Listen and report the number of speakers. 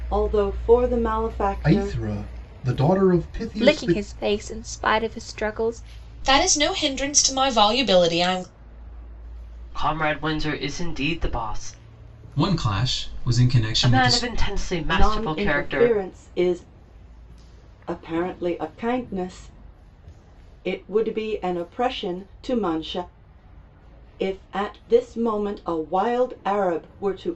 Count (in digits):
6